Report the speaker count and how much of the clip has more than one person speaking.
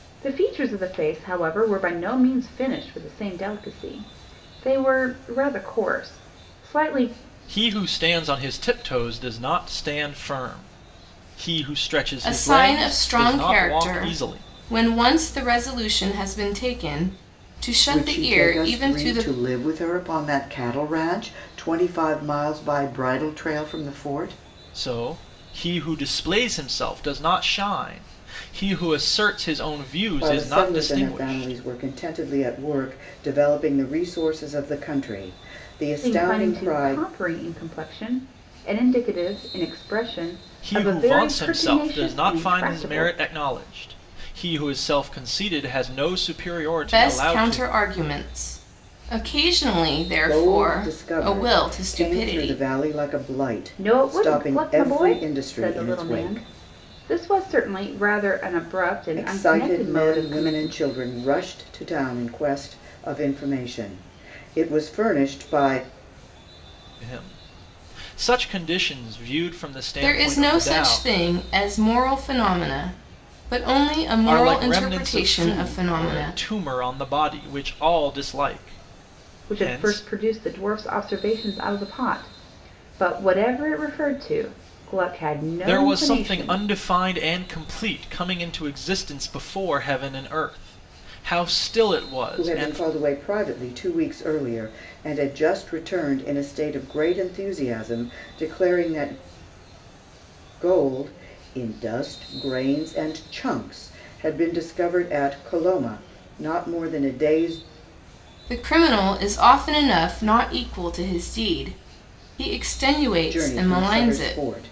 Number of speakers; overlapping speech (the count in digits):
4, about 20%